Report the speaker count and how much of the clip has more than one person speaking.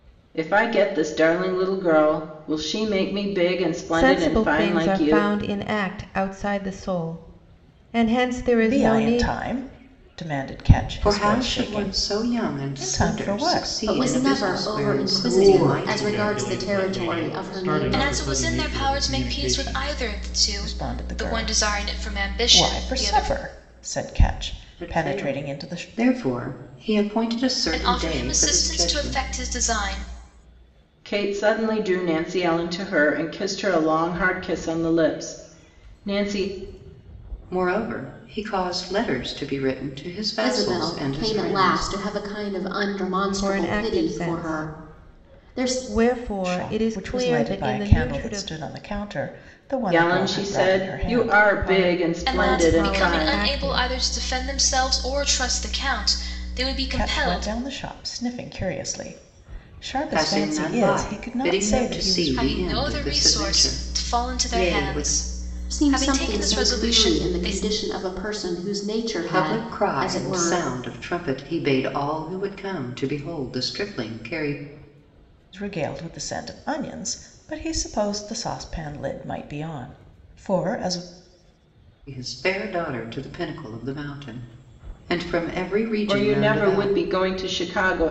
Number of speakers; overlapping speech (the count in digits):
7, about 42%